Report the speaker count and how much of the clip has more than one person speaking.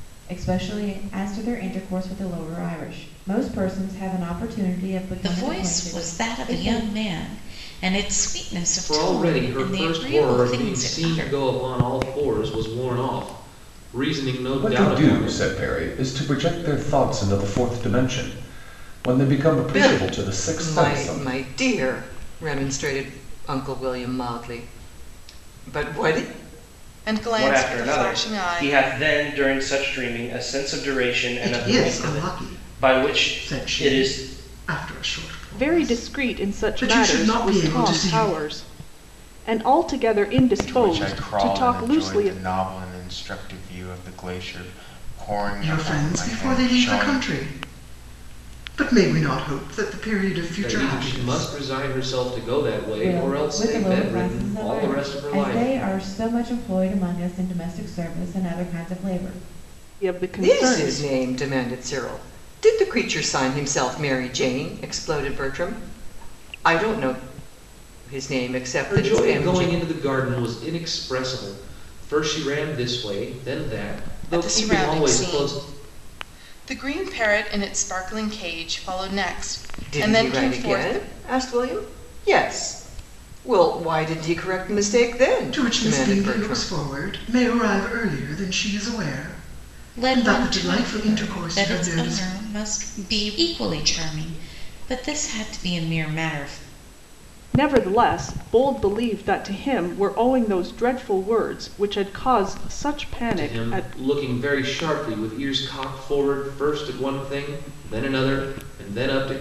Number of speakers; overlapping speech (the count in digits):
10, about 27%